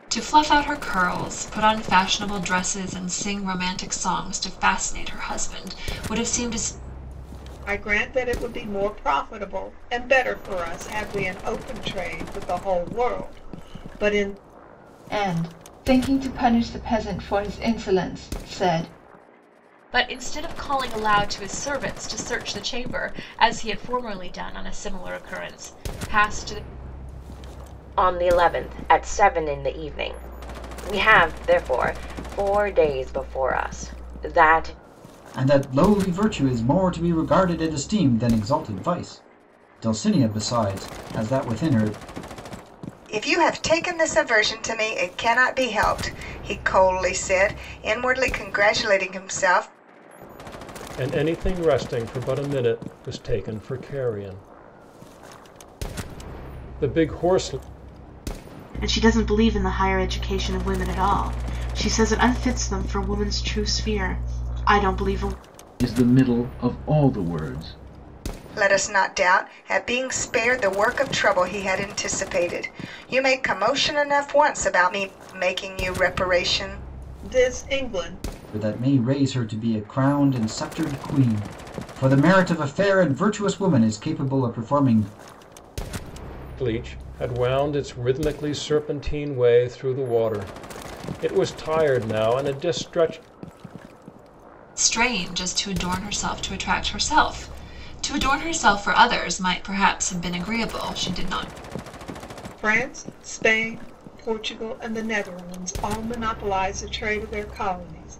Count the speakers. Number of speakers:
10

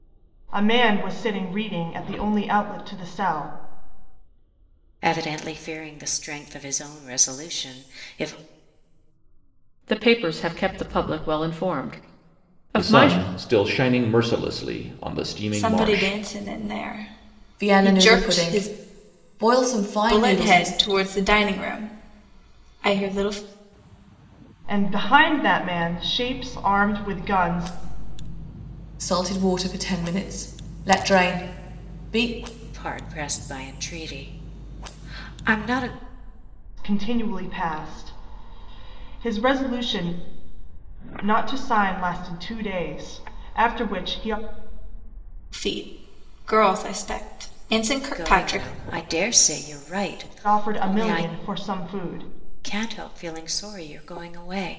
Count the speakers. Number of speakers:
6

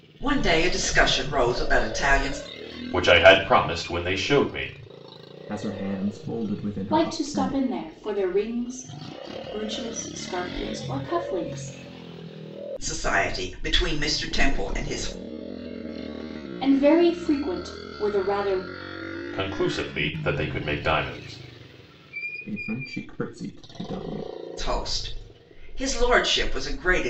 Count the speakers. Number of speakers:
4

